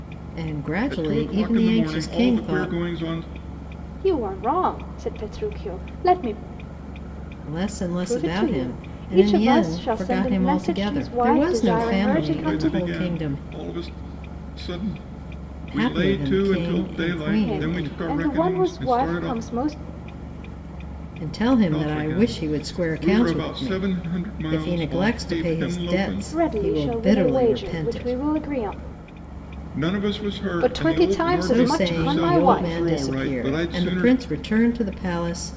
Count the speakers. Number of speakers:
3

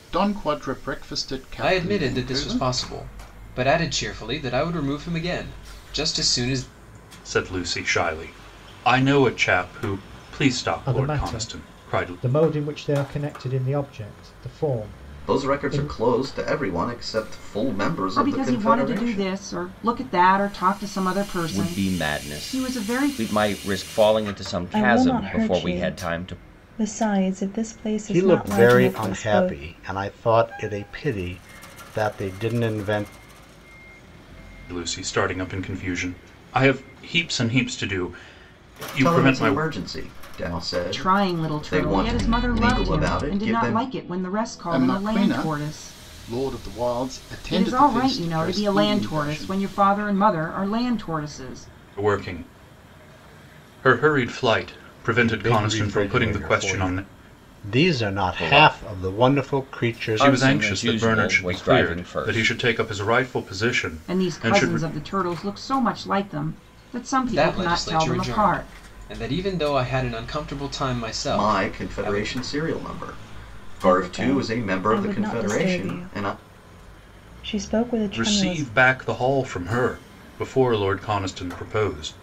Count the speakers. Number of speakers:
9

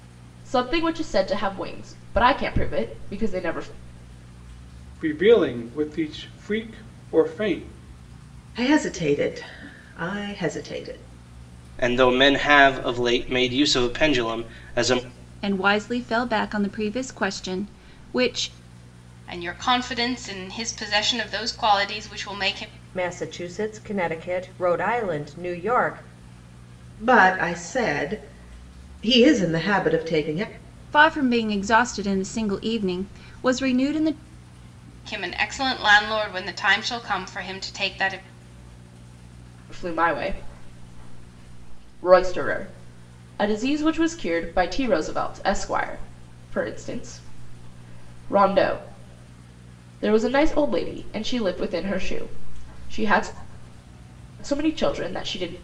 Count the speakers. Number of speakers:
7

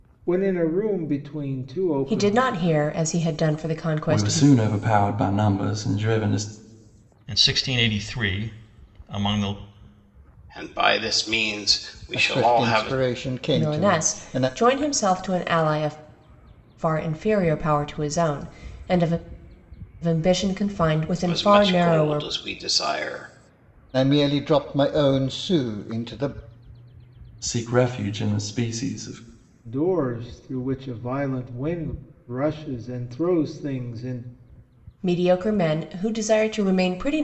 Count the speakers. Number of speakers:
6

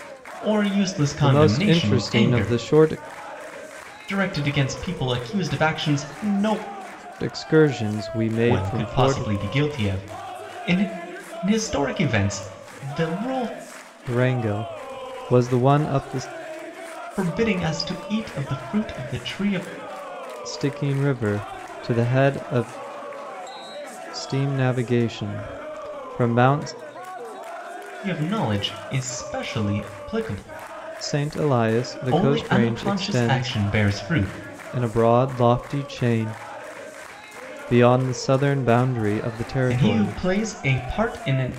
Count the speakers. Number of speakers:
2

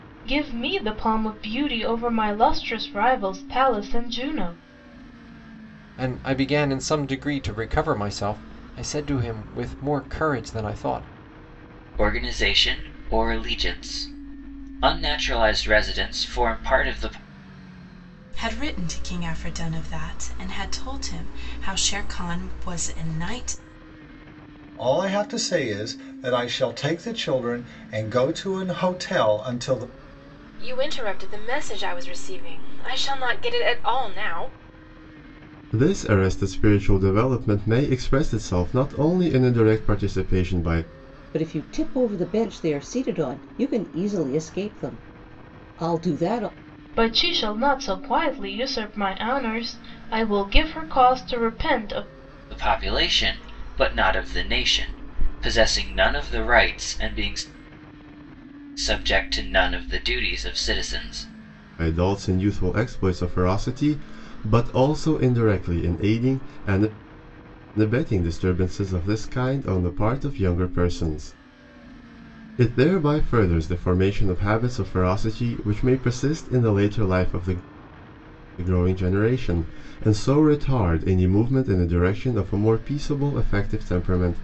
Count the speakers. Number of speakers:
8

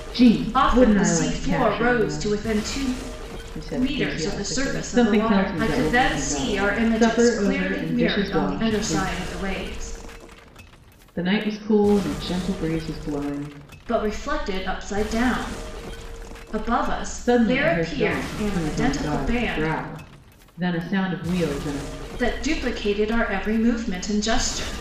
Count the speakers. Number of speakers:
2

